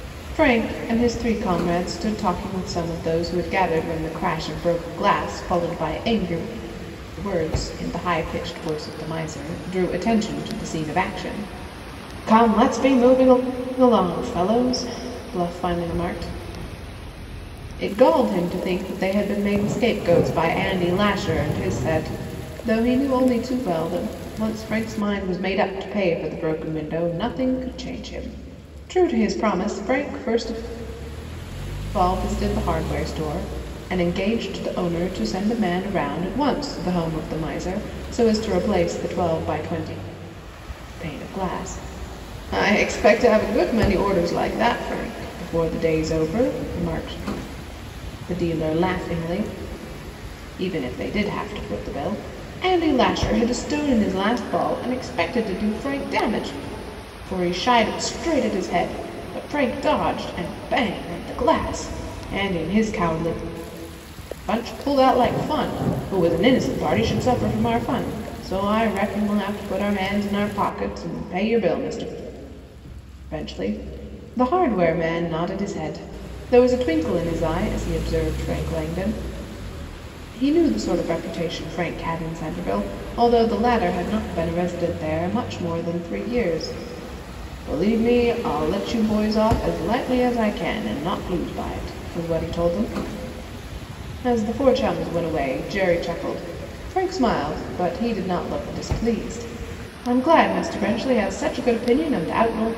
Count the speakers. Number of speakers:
1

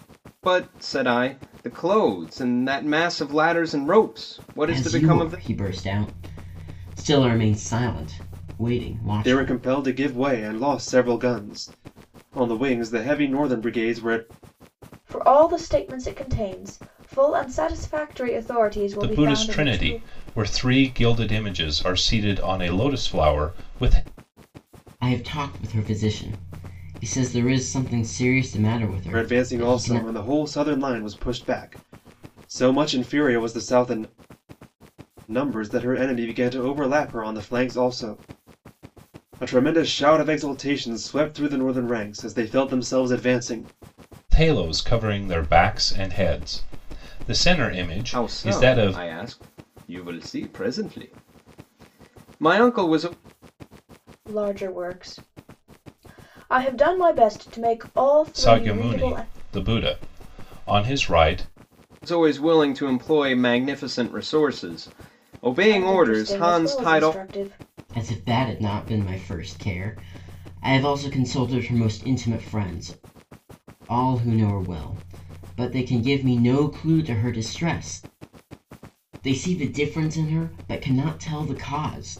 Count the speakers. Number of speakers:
5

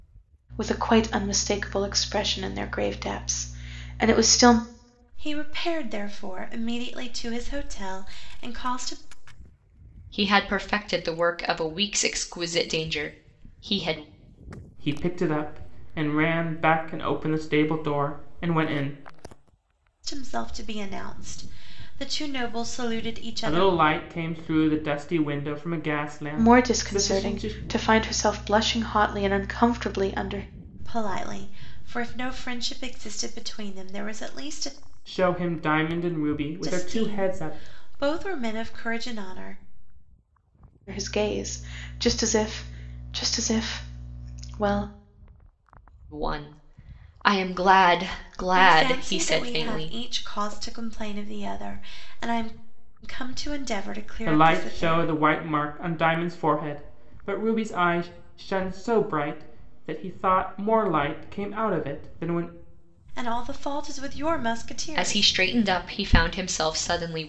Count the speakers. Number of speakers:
4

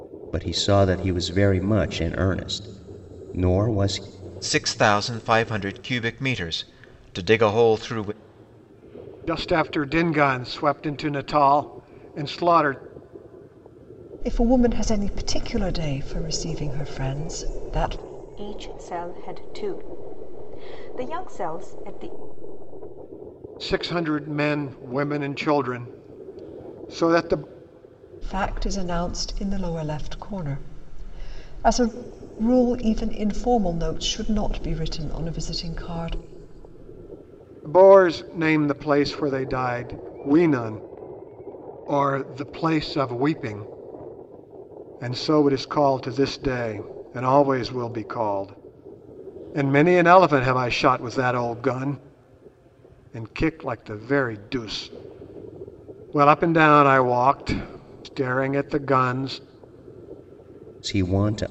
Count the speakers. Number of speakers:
5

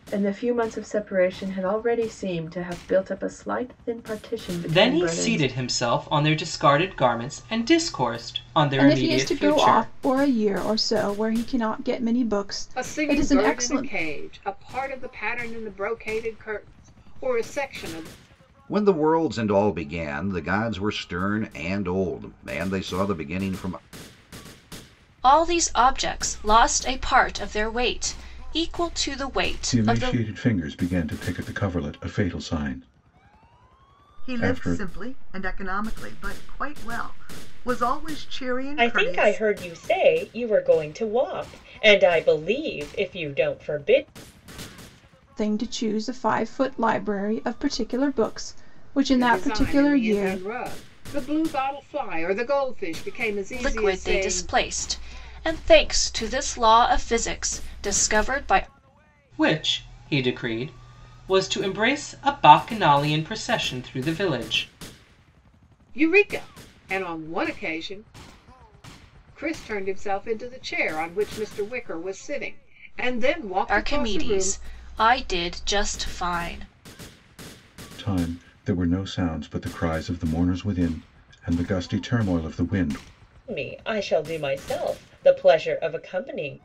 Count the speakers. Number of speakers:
9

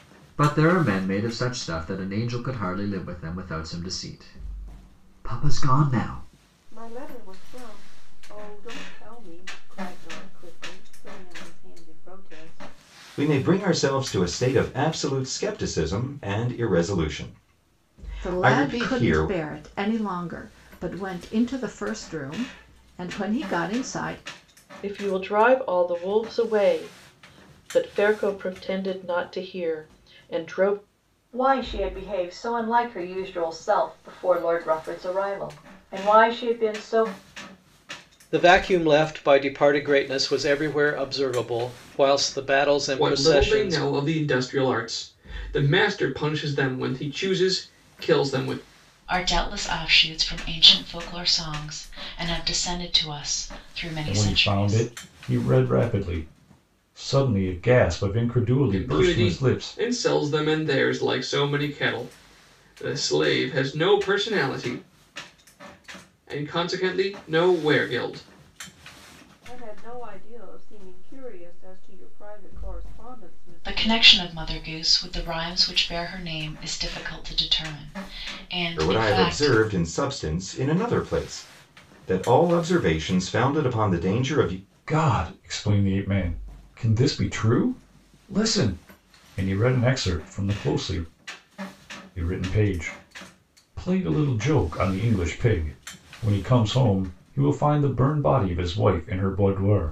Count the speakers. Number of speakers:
10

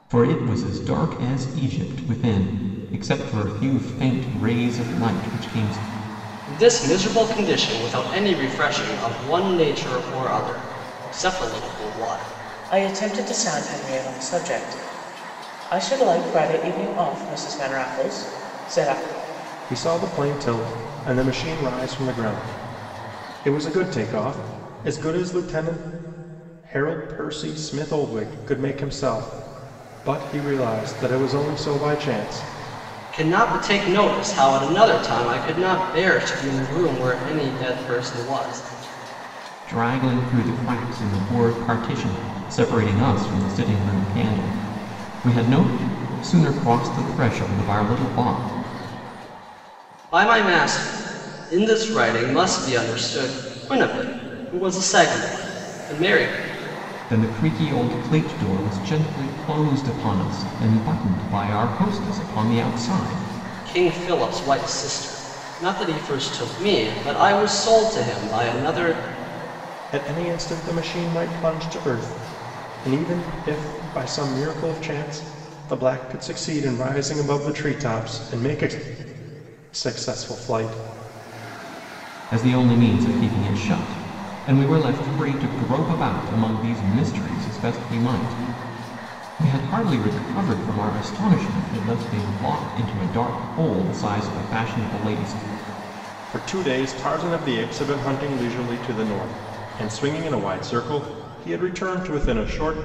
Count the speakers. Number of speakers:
4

